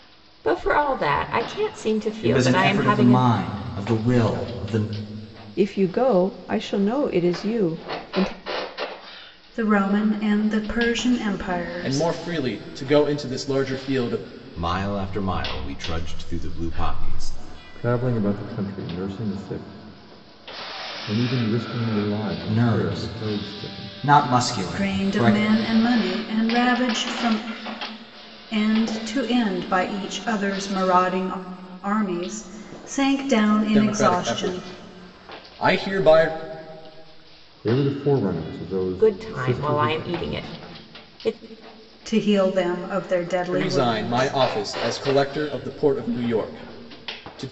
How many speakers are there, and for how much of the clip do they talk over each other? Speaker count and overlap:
seven, about 14%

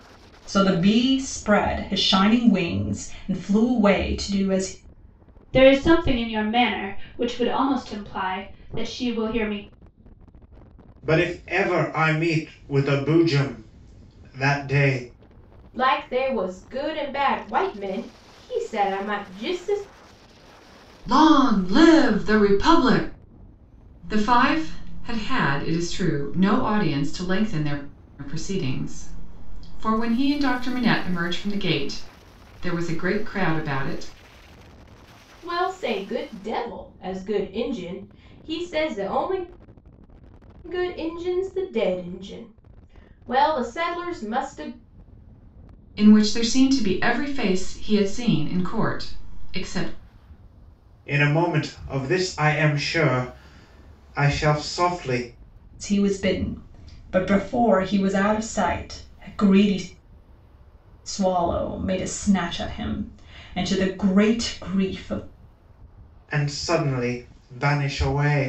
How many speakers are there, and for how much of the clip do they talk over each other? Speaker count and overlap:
five, no overlap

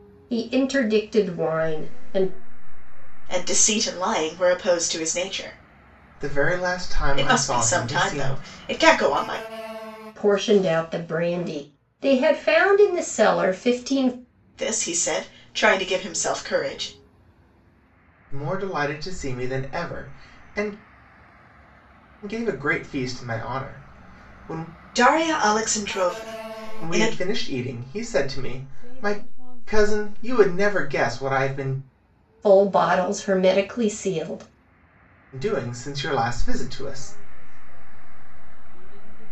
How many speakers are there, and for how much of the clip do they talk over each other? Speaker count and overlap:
four, about 14%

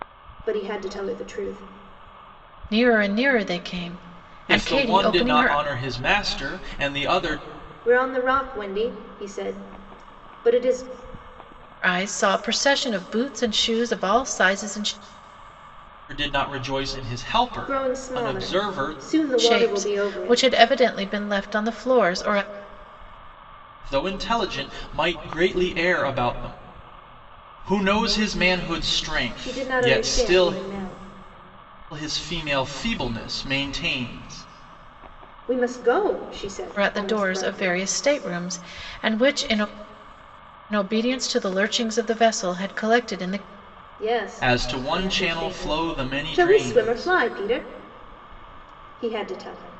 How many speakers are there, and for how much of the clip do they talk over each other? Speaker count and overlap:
three, about 16%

